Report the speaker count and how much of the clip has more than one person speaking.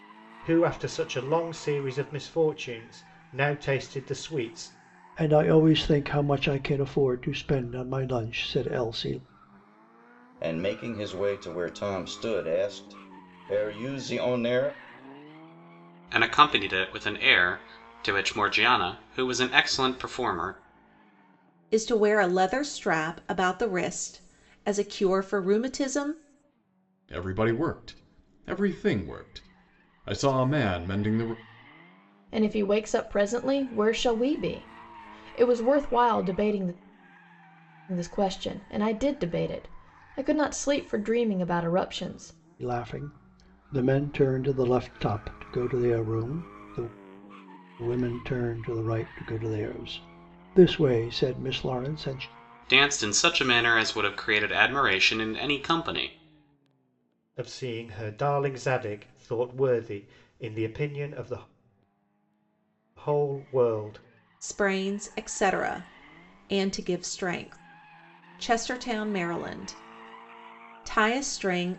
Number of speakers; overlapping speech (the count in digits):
7, no overlap